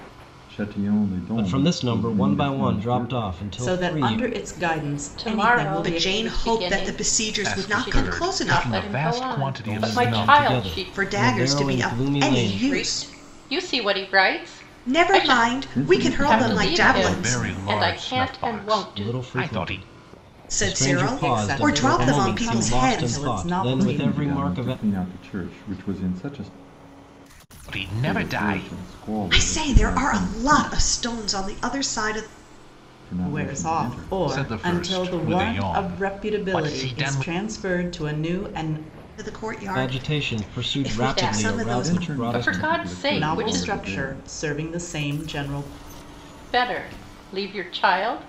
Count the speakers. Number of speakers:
six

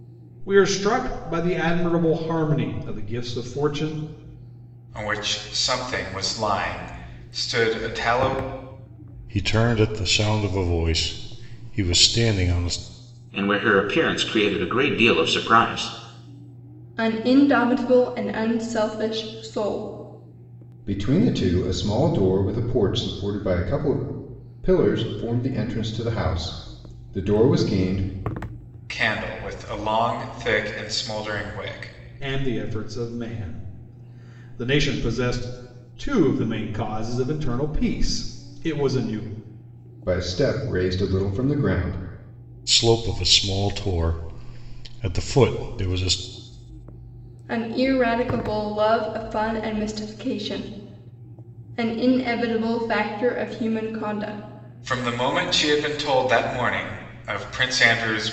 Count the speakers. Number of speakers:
six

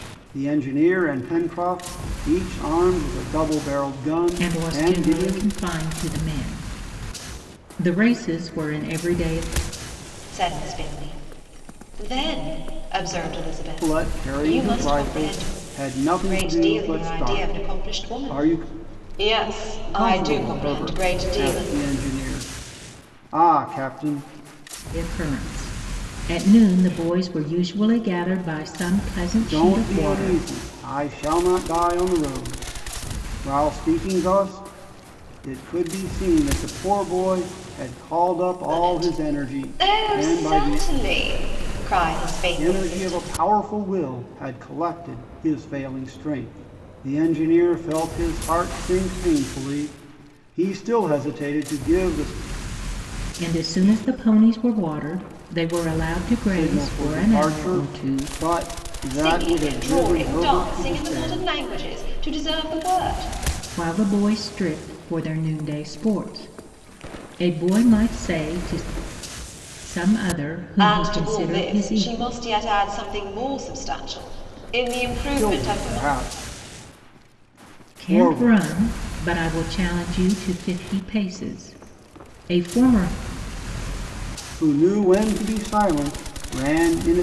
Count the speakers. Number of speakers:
three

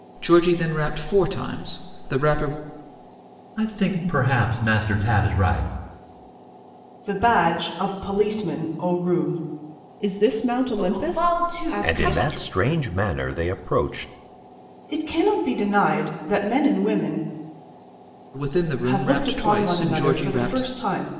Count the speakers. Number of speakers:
six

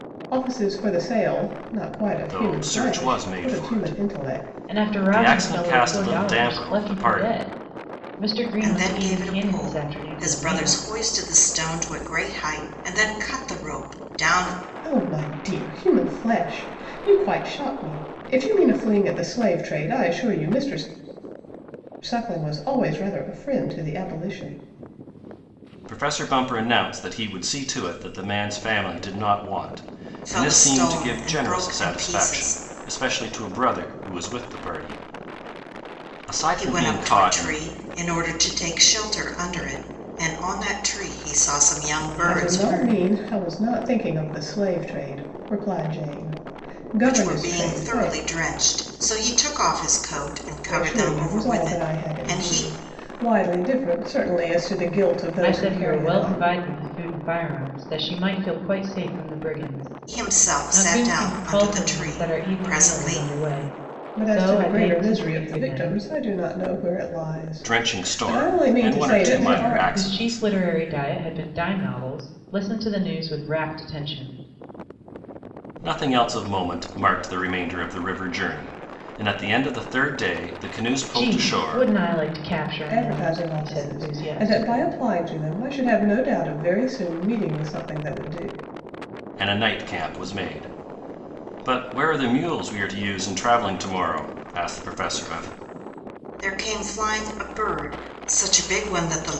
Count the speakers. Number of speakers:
four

